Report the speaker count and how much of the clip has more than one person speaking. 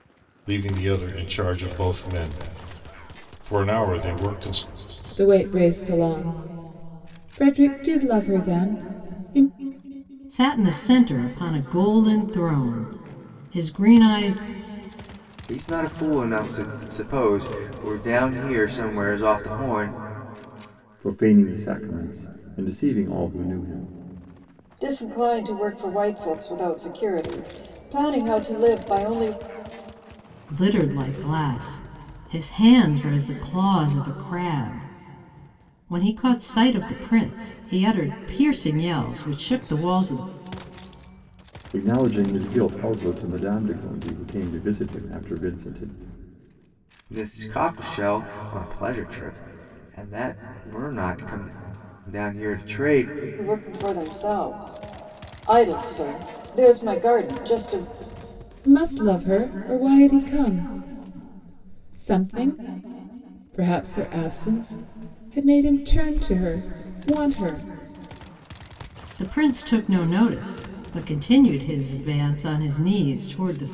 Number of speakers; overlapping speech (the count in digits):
6, no overlap